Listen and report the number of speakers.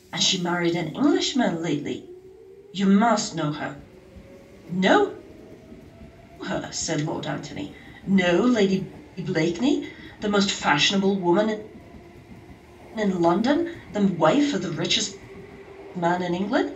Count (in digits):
1